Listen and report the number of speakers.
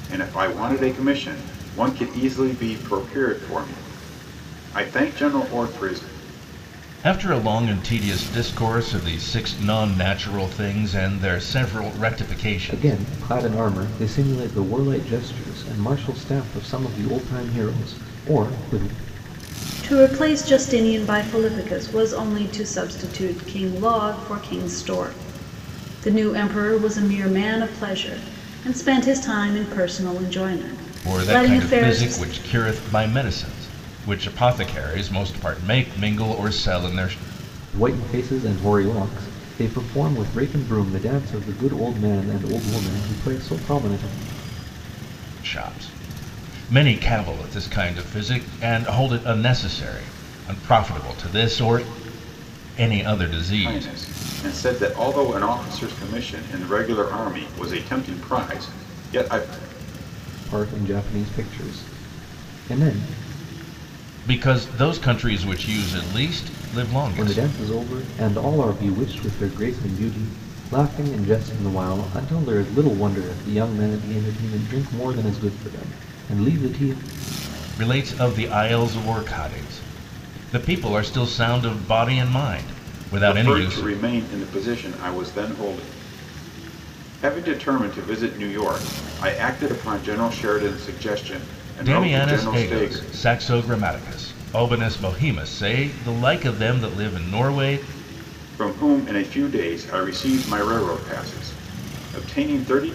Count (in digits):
4